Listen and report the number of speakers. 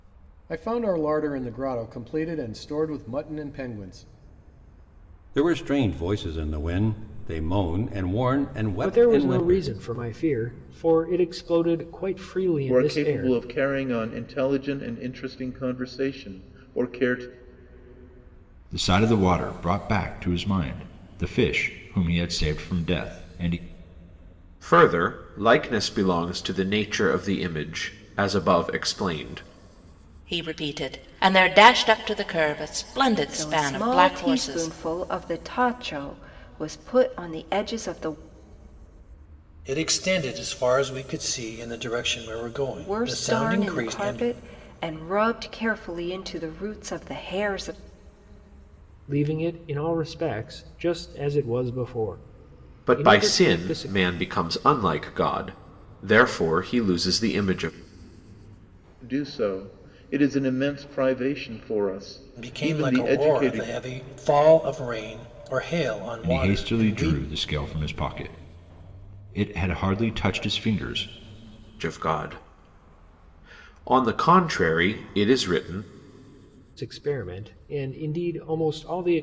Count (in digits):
9